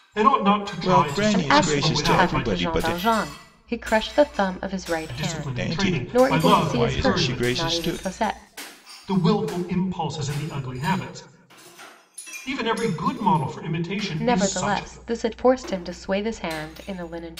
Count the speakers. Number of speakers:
3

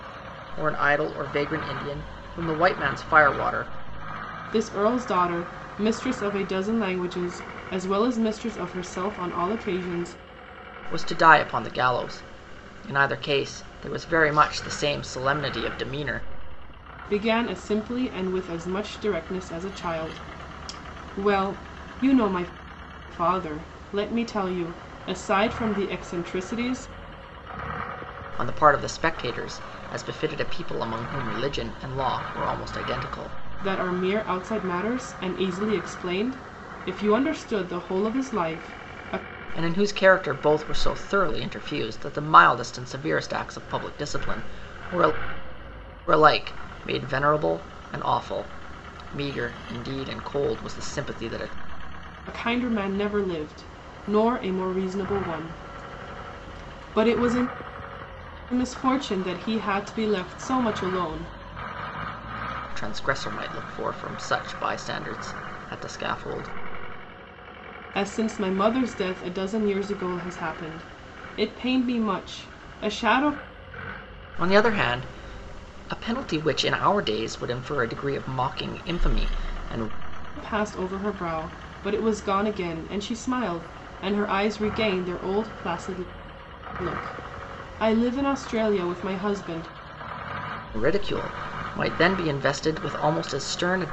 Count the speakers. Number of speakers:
2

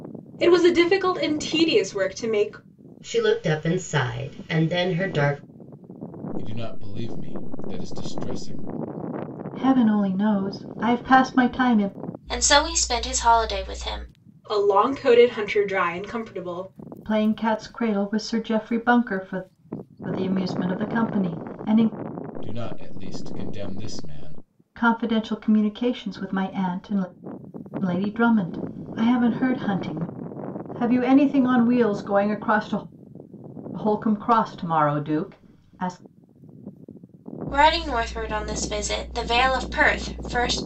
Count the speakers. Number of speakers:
5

